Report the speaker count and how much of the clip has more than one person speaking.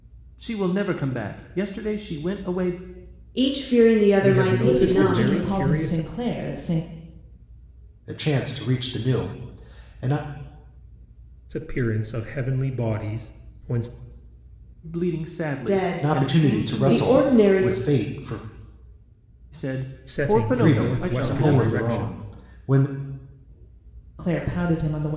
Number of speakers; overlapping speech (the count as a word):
five, about 24%